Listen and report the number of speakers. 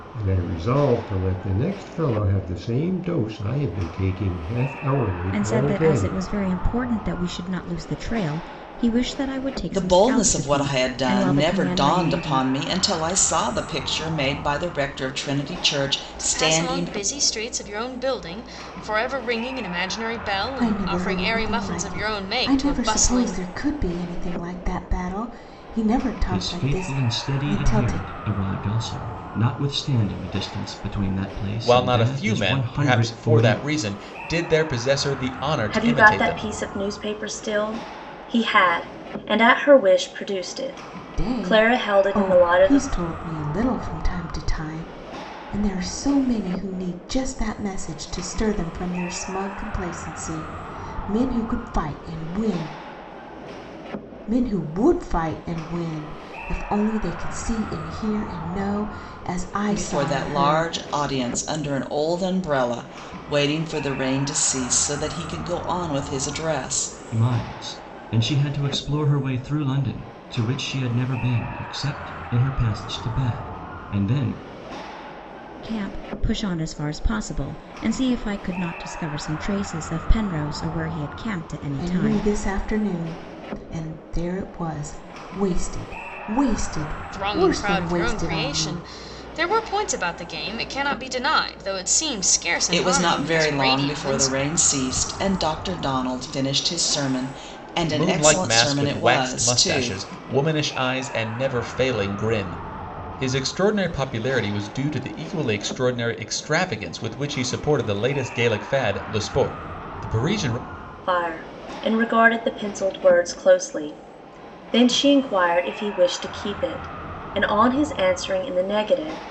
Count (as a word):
eight